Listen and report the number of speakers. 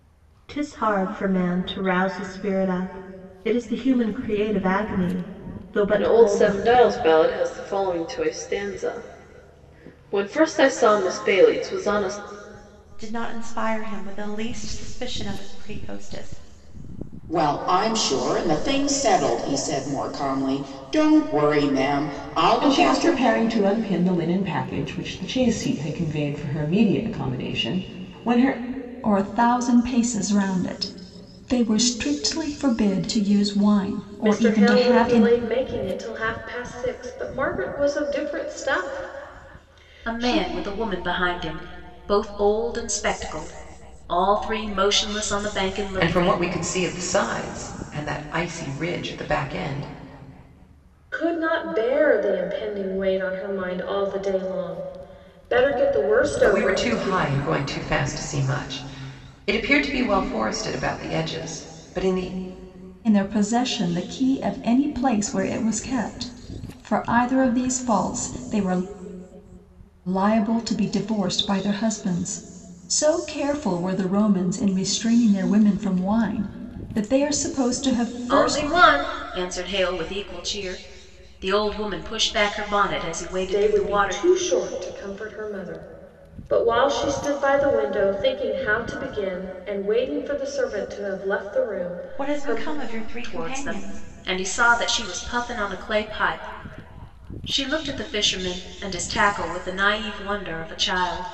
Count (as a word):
nine